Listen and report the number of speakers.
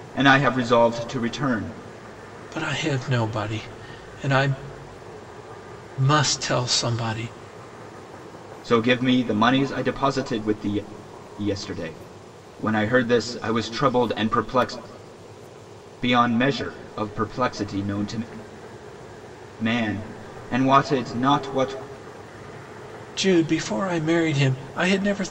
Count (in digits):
2